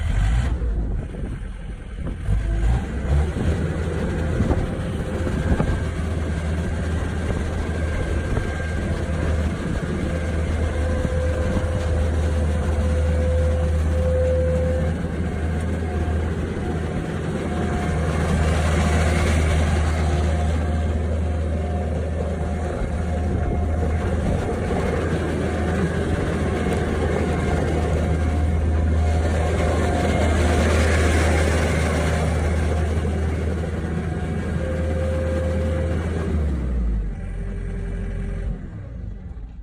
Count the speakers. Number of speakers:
zero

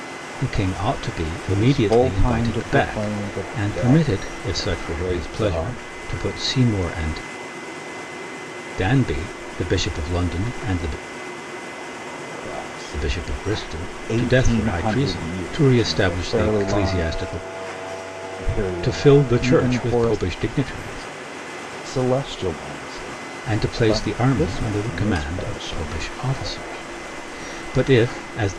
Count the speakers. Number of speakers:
two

